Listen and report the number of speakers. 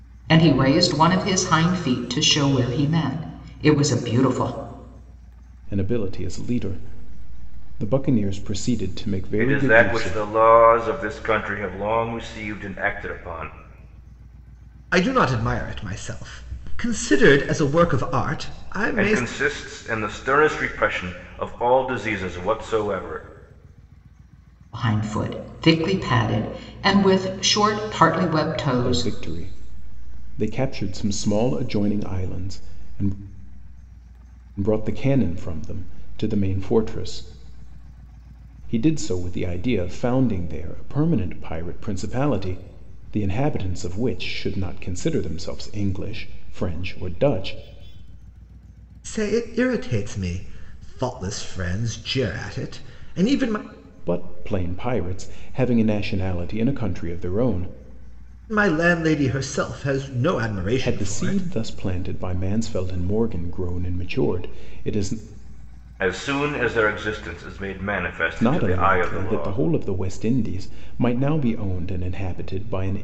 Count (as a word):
four